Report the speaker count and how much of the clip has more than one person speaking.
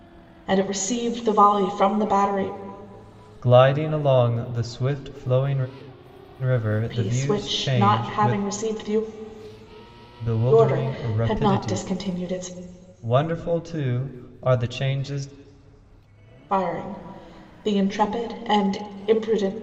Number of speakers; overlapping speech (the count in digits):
2, about 15%